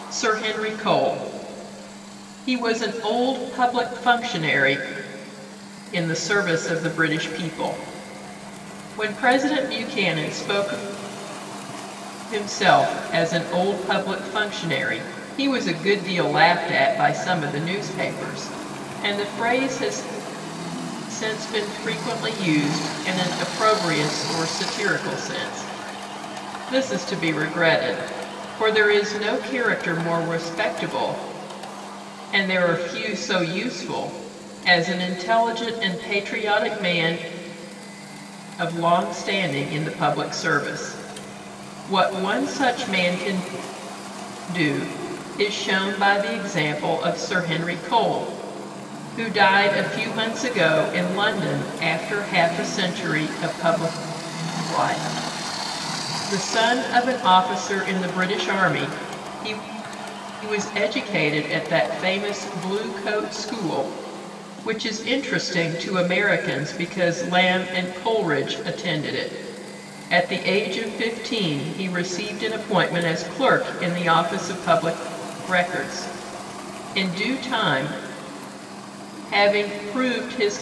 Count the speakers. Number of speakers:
one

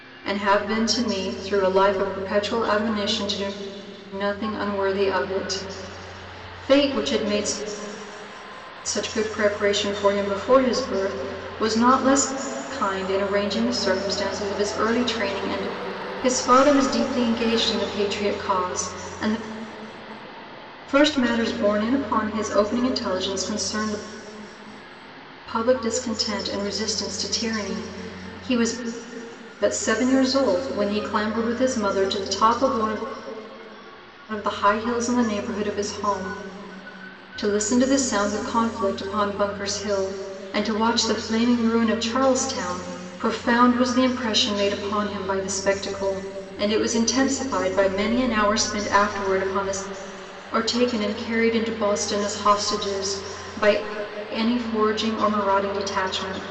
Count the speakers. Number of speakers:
one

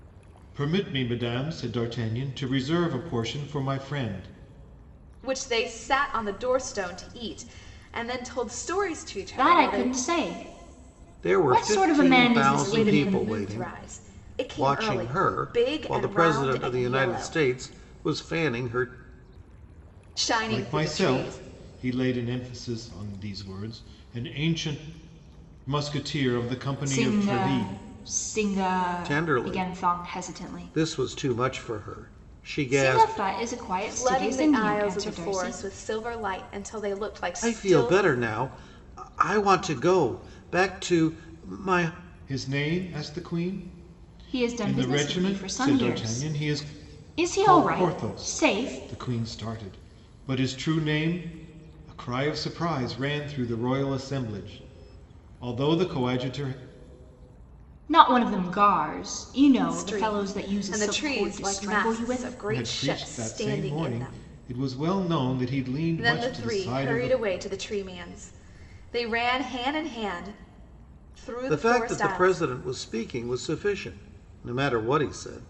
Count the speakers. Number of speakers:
four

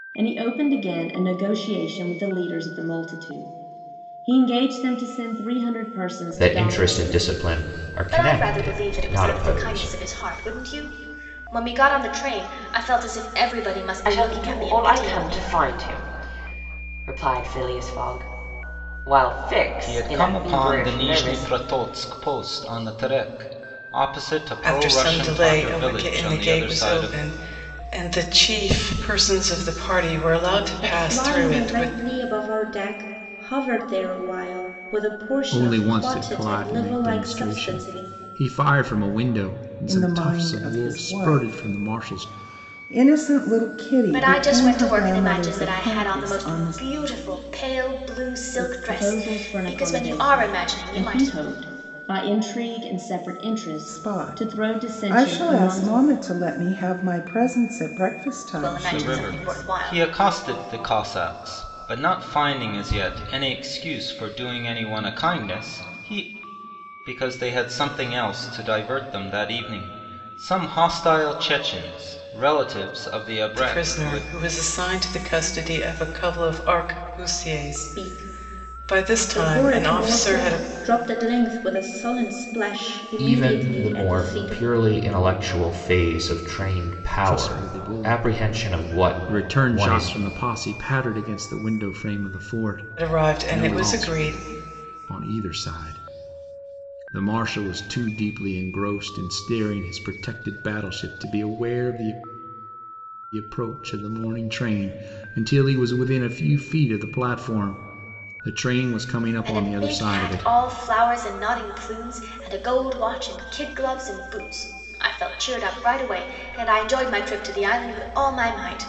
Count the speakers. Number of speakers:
nine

